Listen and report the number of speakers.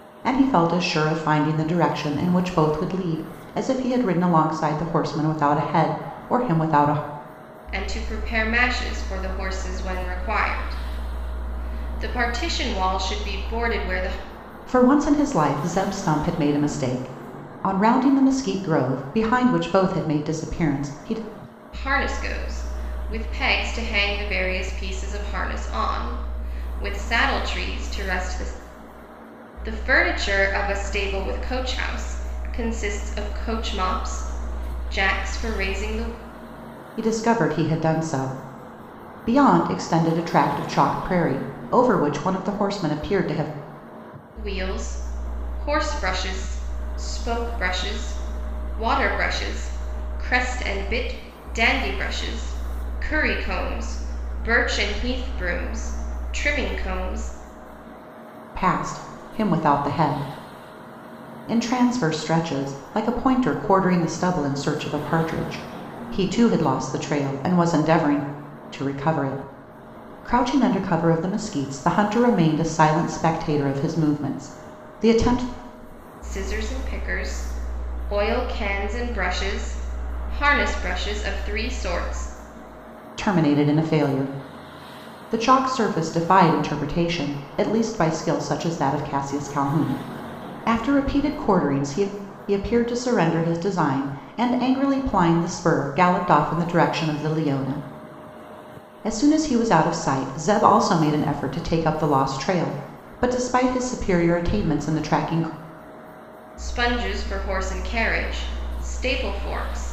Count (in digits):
2